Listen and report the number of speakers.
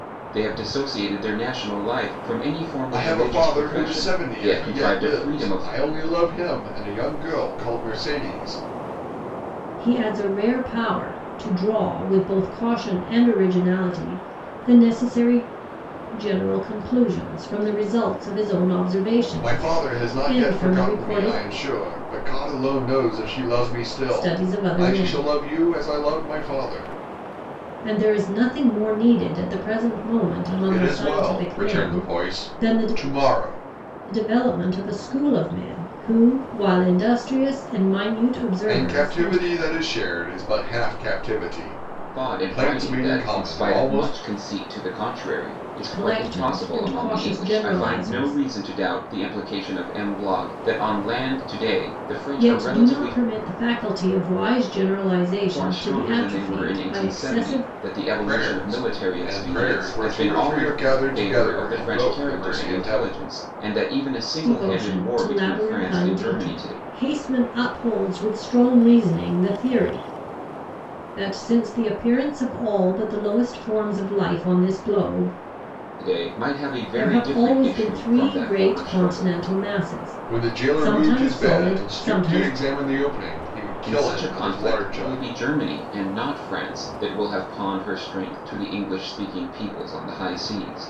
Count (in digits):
3